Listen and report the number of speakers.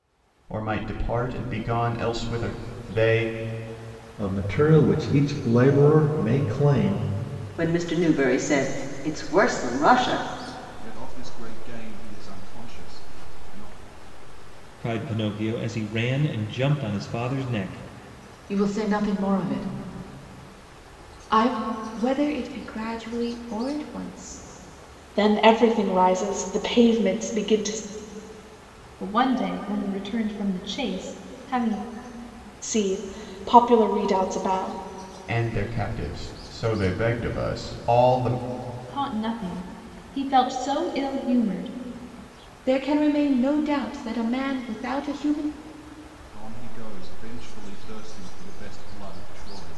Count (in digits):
9